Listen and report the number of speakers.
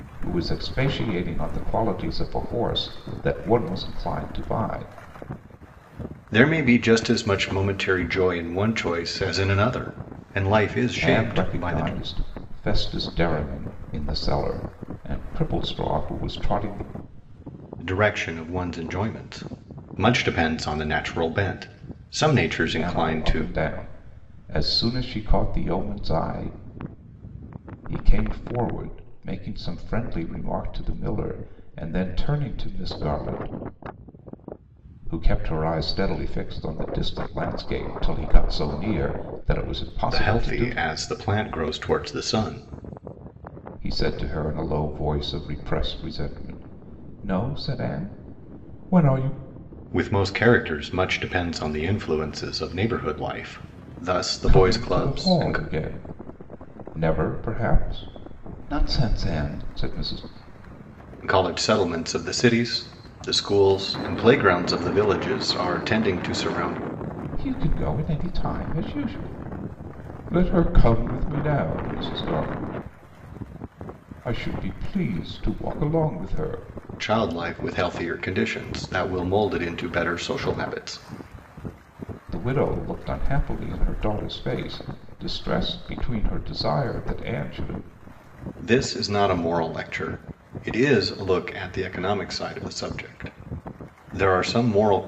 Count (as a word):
two